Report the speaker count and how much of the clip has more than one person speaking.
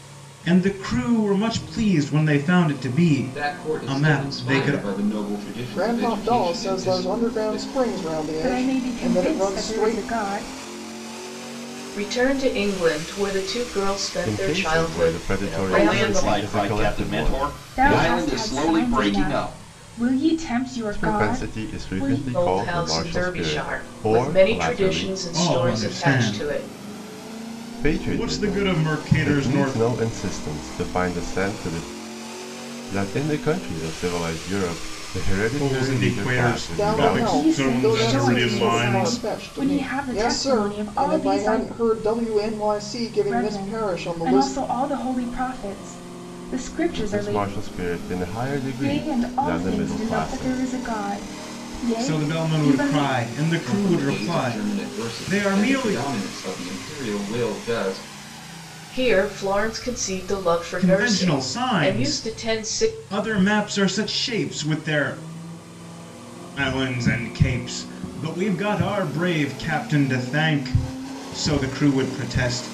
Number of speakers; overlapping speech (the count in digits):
7, about 47%